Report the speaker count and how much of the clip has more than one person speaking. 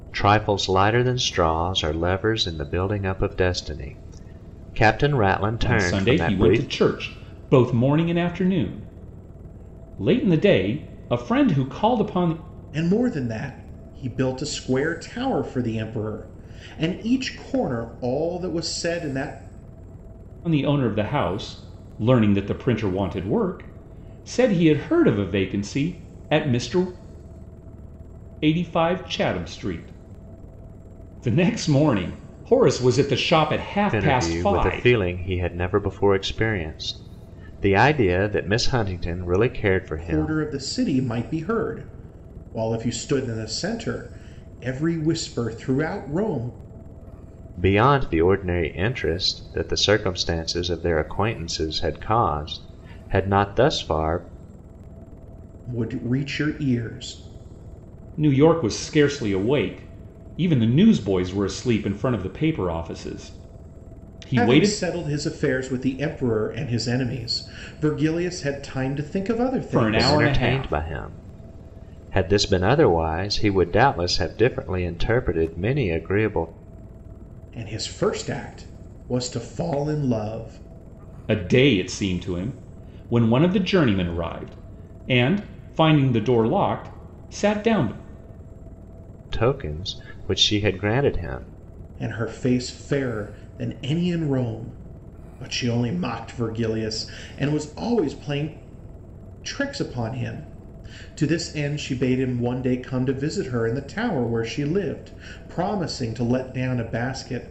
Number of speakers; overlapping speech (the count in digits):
3, about 4%